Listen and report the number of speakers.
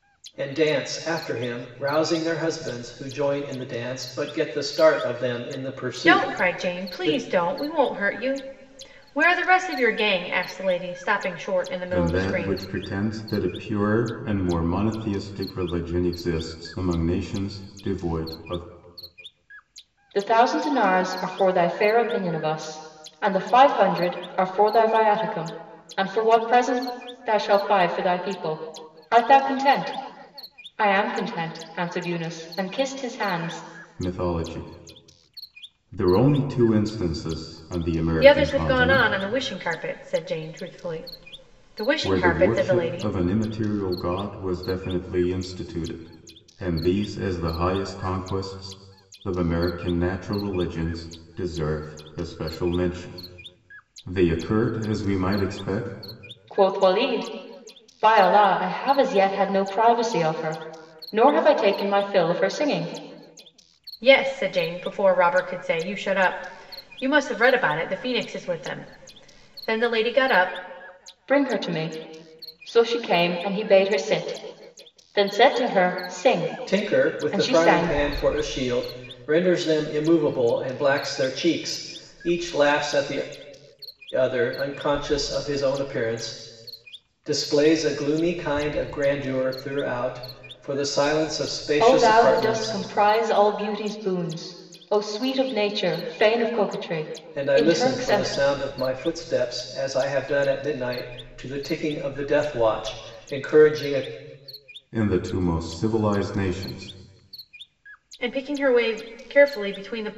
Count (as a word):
four